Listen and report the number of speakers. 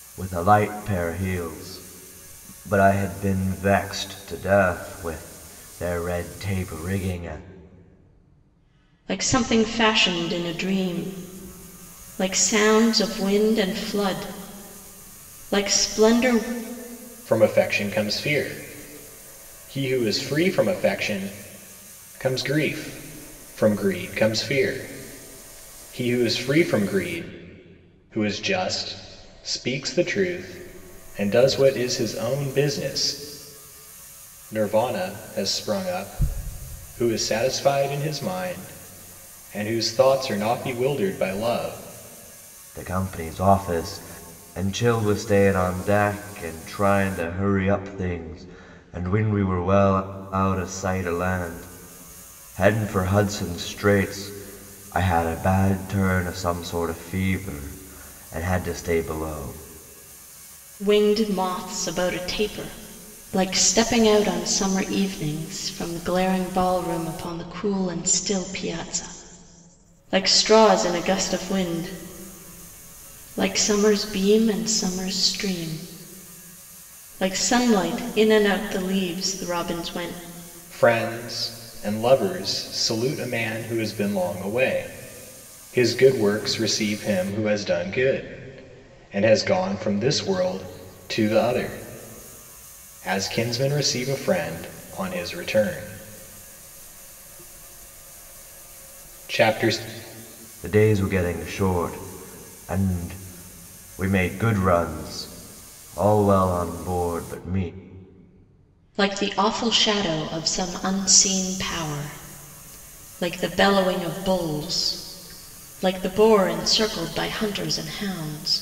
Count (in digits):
3